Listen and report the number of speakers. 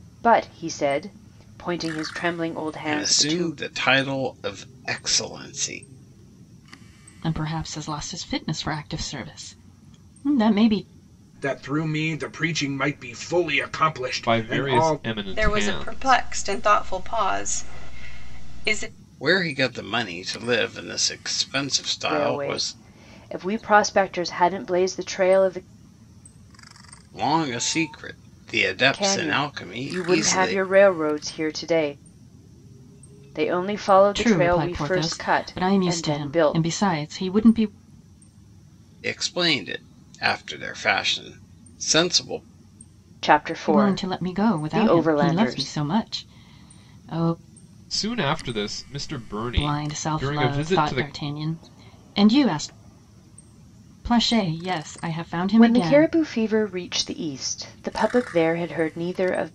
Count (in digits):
6